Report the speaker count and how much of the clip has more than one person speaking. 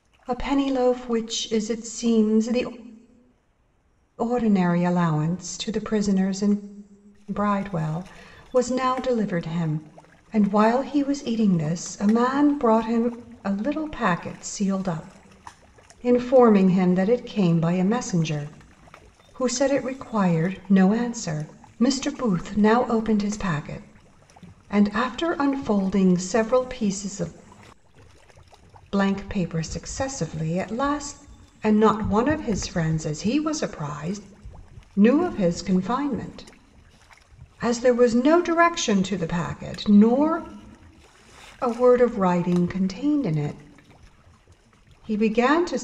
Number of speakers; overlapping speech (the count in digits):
1, no overlap